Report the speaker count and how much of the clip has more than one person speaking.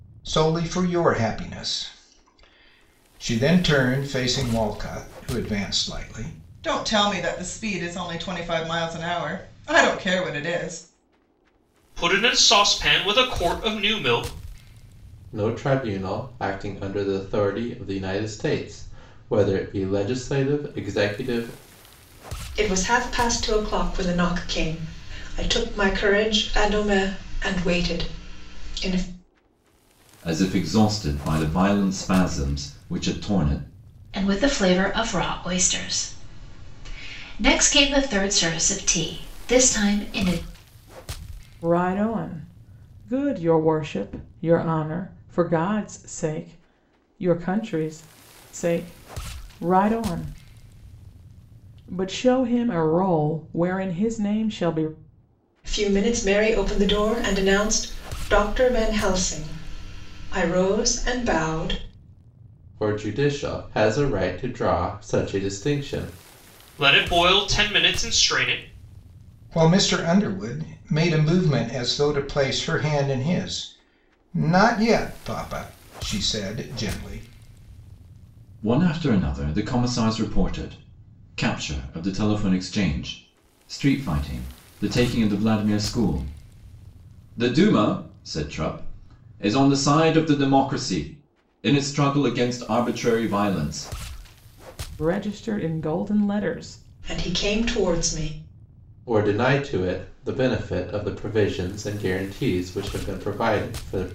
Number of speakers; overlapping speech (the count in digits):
8, no overlap